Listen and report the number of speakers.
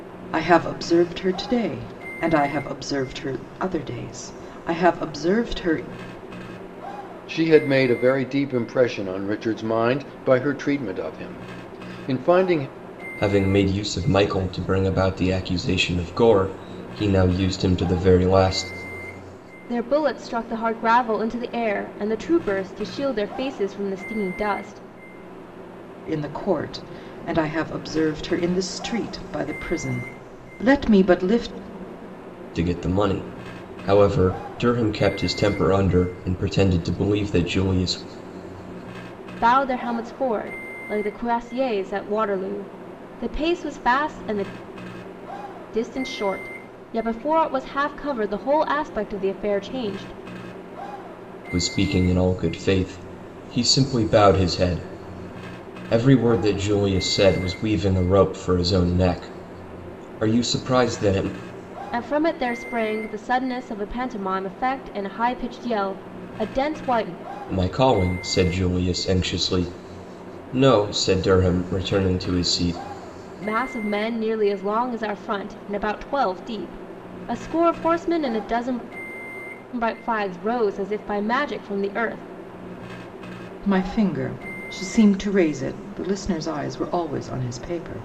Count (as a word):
four